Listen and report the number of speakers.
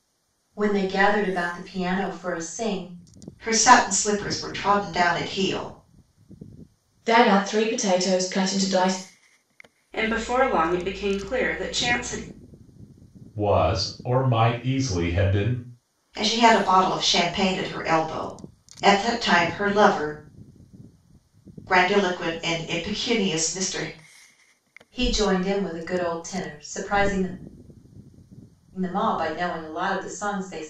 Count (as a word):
five